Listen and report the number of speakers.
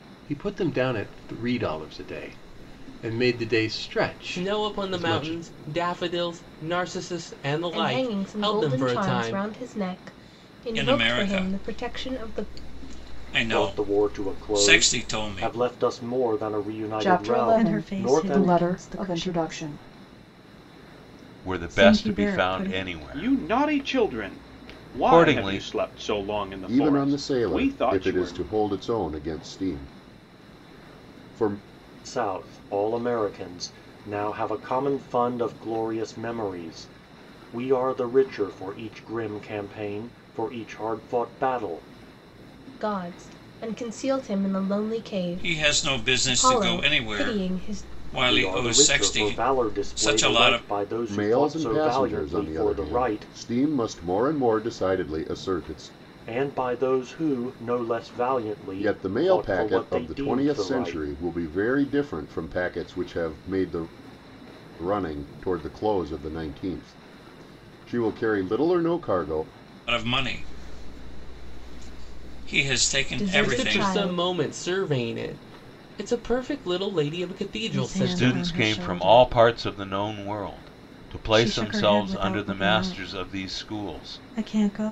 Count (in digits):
10